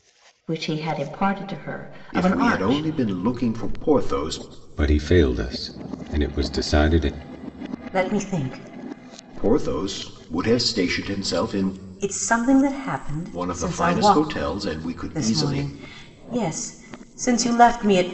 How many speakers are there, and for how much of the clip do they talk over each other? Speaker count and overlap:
4, about 13%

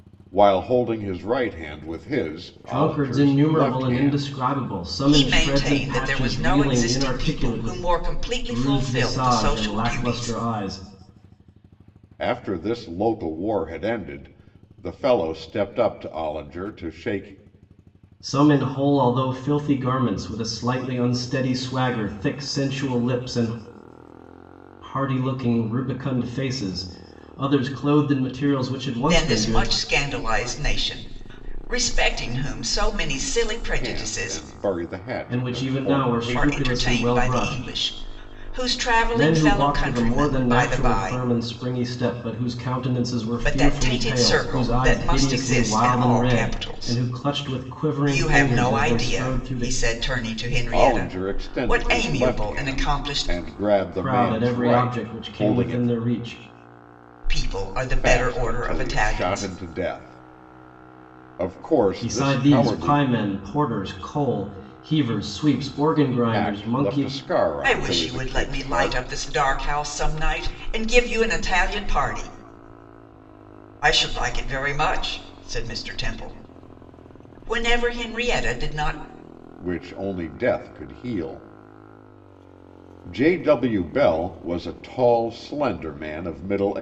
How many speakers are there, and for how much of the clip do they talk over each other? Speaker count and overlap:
3, about 32%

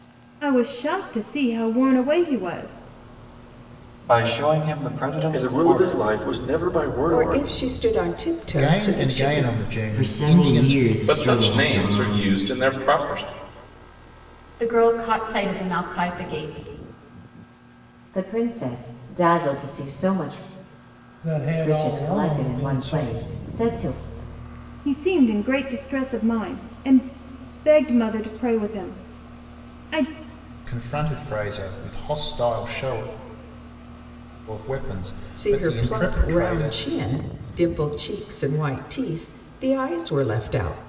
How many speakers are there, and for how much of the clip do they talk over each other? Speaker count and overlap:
10, about 18%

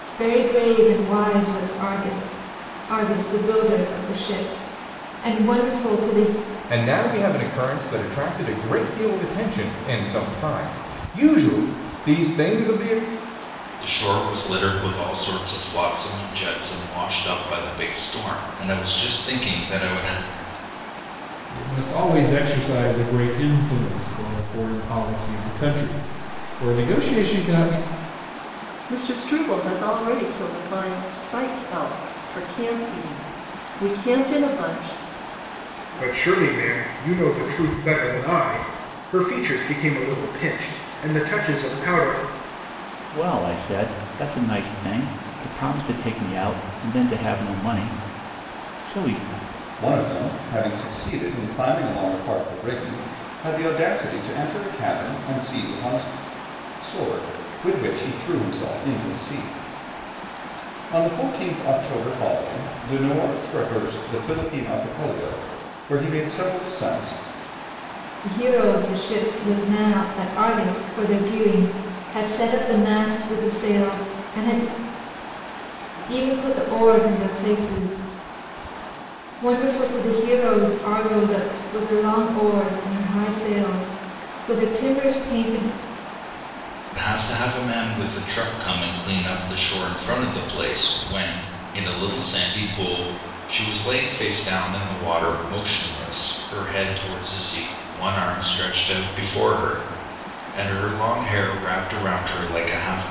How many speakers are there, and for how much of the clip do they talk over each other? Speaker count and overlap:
8, no overlap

